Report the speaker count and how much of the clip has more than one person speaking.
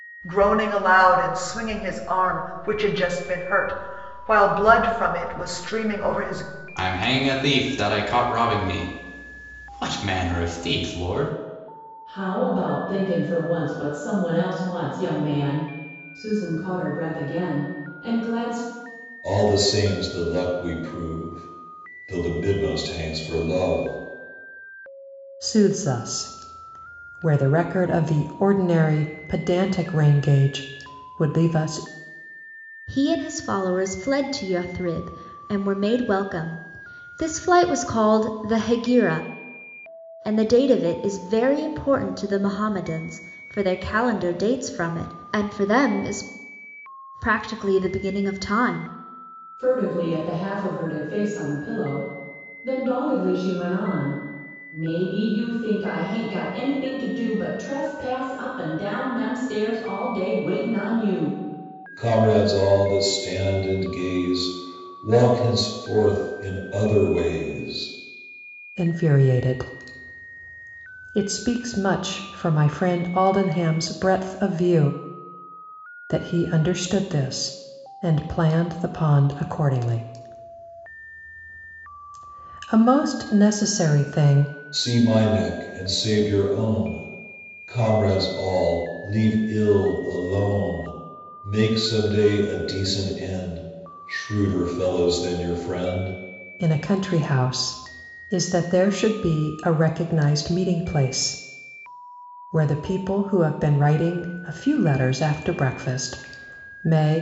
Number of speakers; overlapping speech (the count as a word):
six, no overlap